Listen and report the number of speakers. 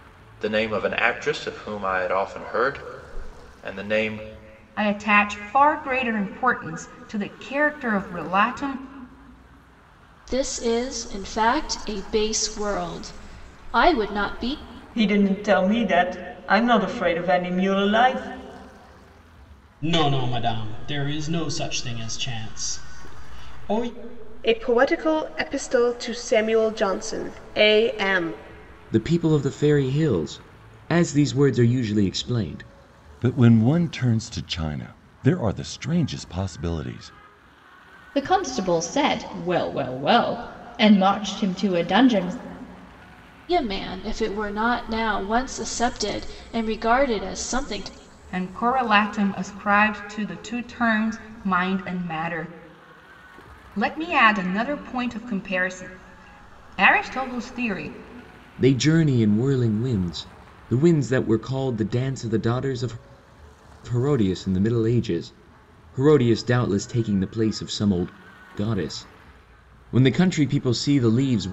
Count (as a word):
nine